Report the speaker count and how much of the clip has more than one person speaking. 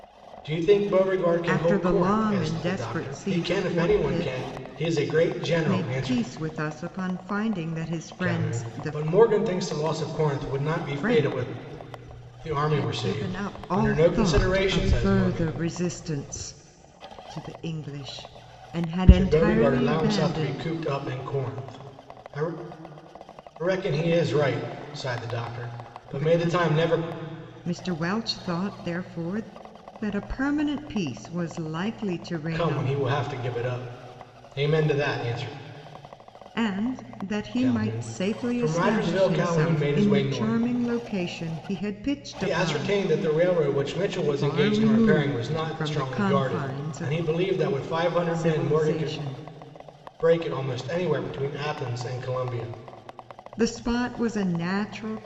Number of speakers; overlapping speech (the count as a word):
two, about 35%